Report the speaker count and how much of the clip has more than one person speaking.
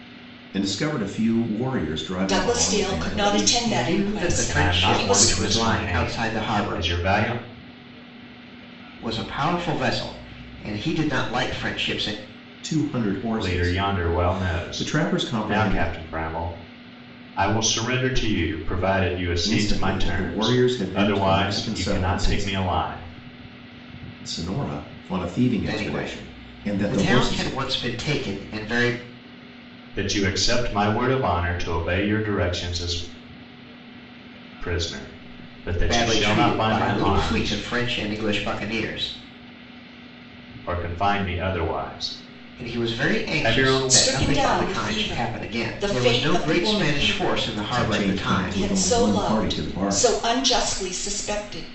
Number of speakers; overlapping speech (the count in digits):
4, about 40%